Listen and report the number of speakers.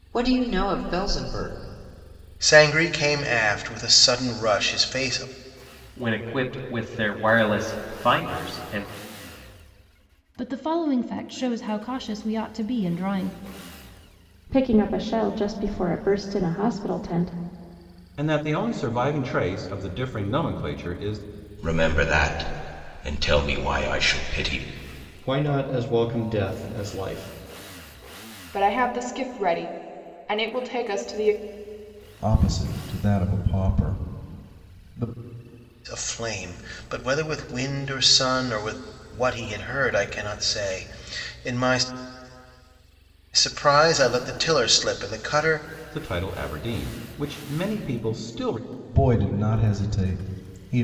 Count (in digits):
10